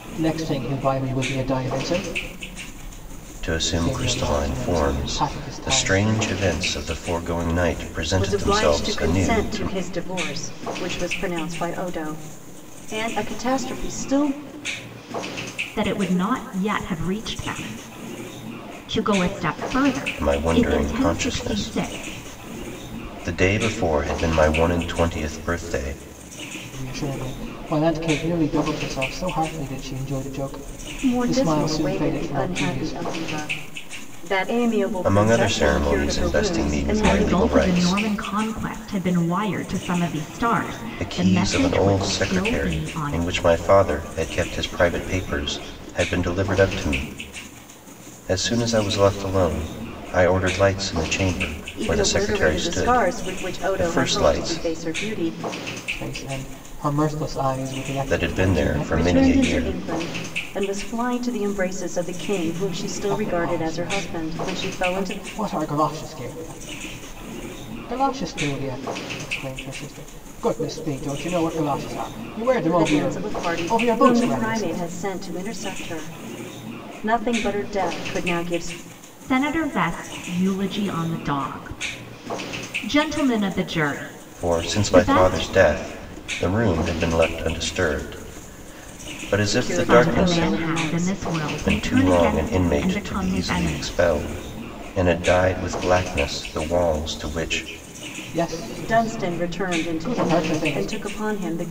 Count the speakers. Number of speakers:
four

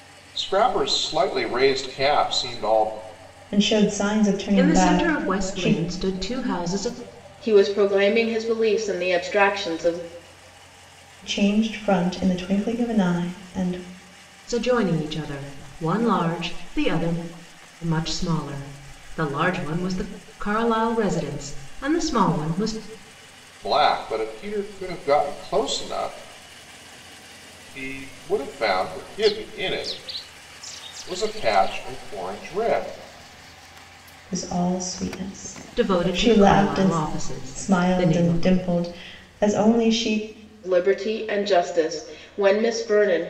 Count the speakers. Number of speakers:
four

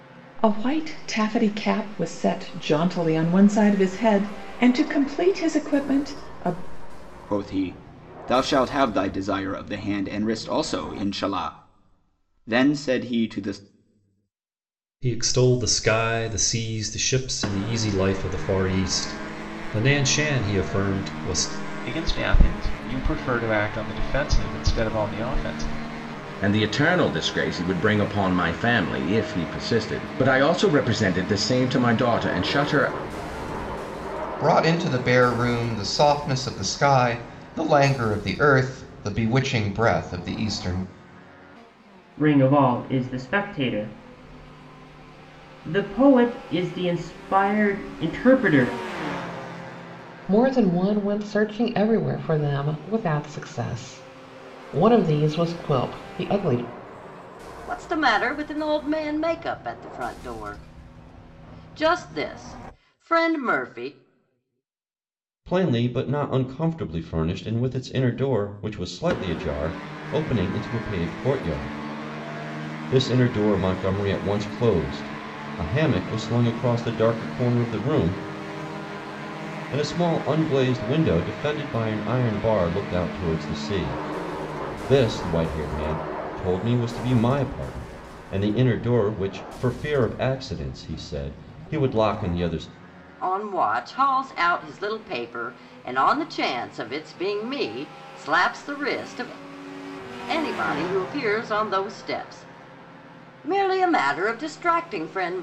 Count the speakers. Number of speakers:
ten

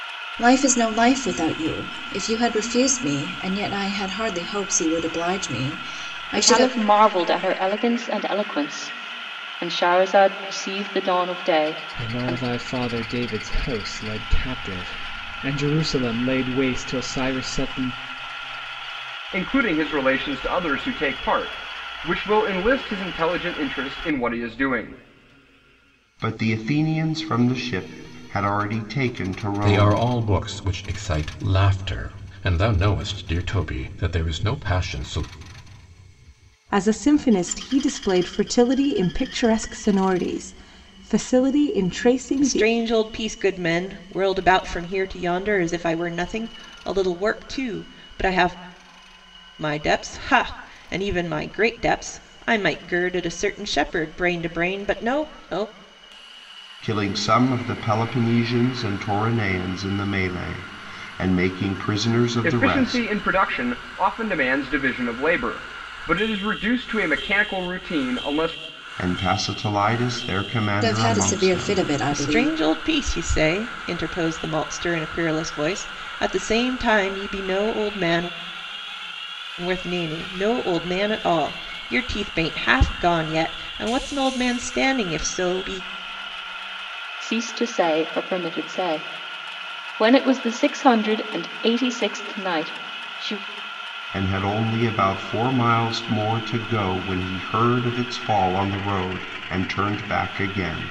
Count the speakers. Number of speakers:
eight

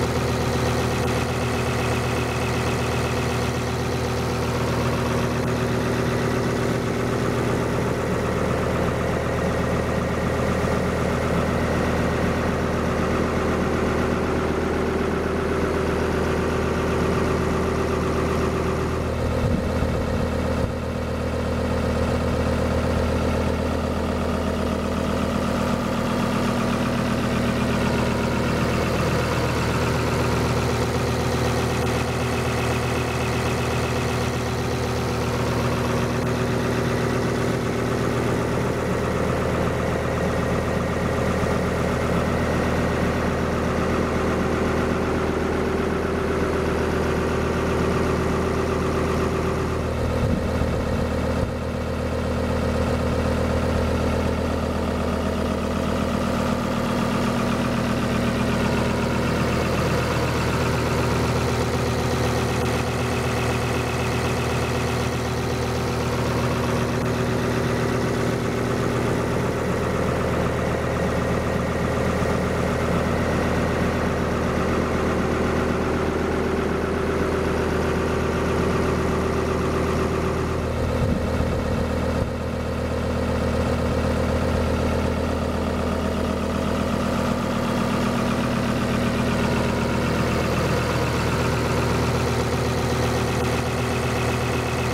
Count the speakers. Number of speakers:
zero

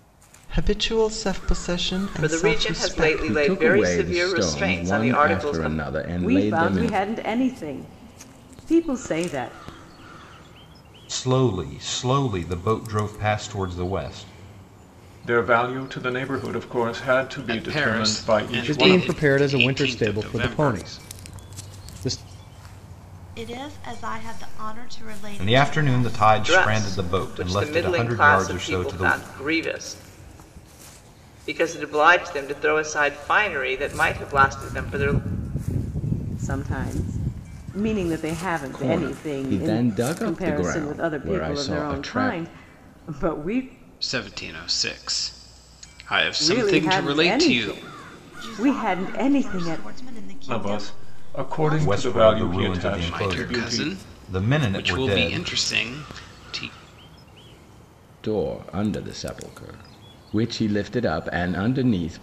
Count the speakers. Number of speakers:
nine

